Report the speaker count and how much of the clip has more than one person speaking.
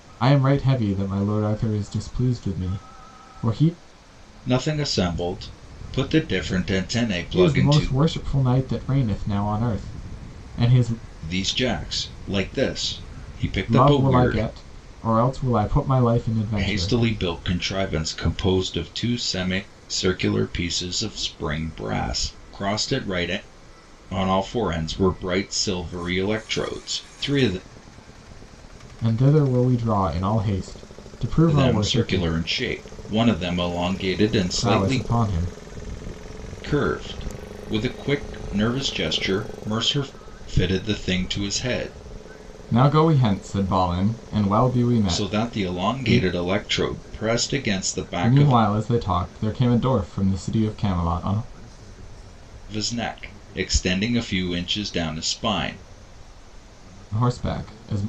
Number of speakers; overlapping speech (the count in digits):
2, about 8%